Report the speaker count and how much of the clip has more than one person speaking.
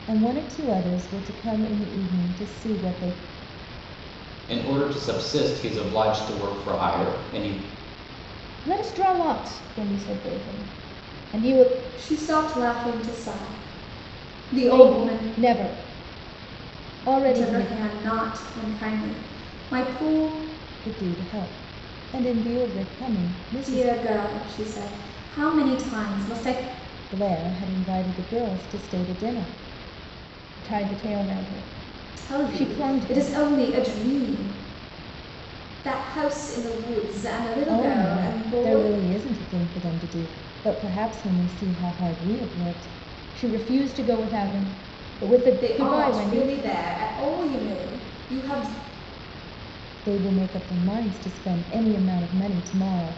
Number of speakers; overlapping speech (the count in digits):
4, about 9%